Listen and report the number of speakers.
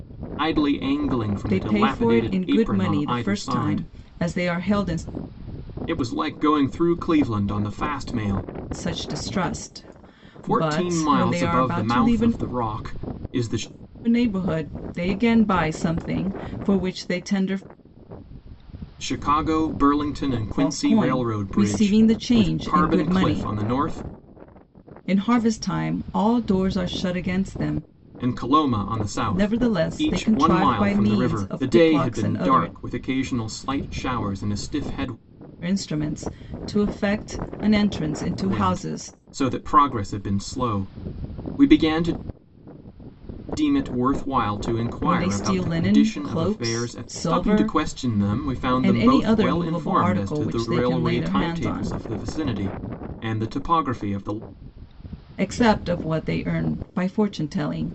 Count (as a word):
two